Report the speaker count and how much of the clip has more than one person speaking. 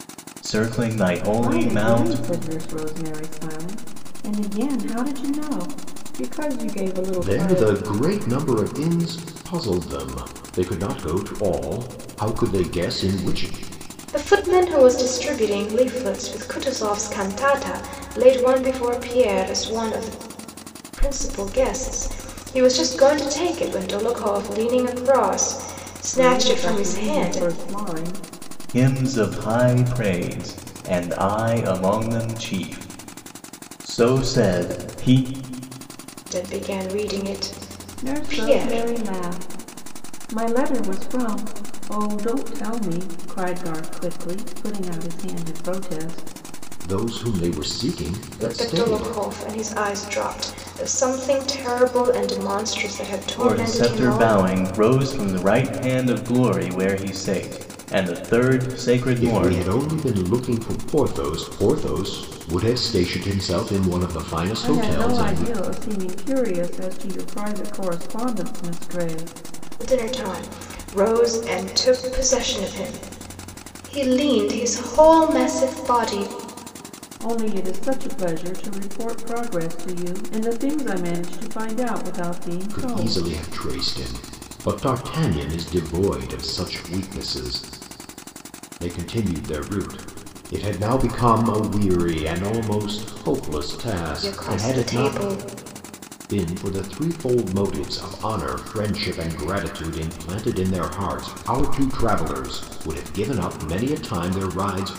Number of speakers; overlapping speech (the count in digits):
4, about 8%